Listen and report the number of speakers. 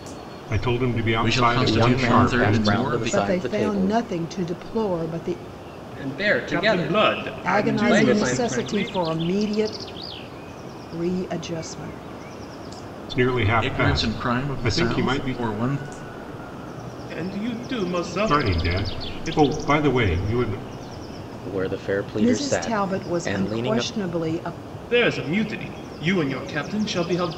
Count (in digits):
6